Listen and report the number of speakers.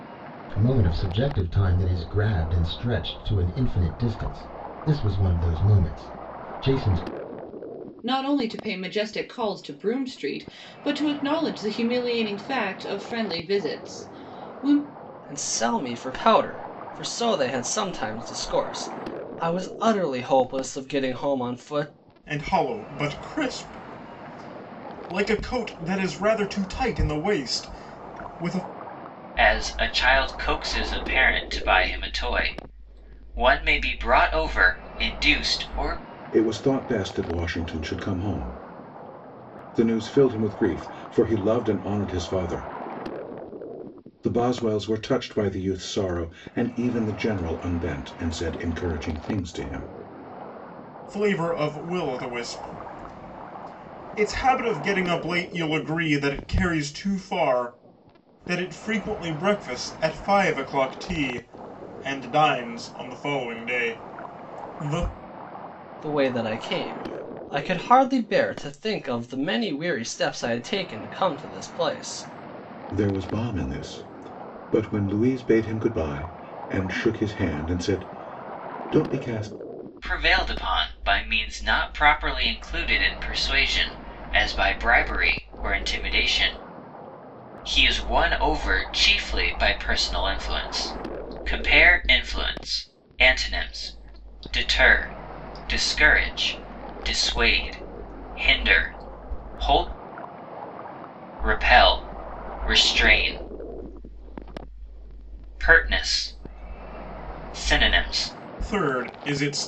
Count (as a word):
six